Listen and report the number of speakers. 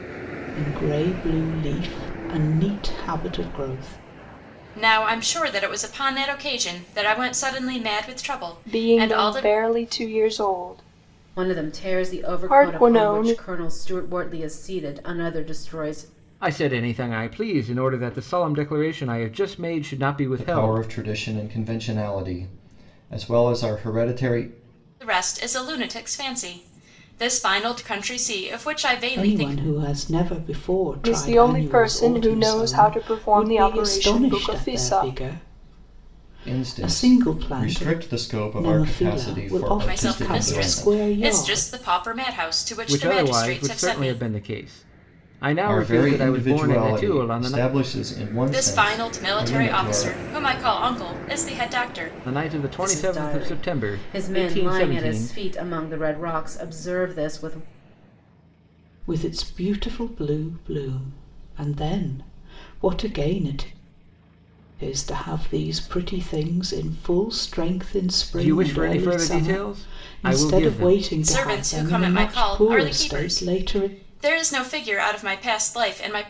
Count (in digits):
6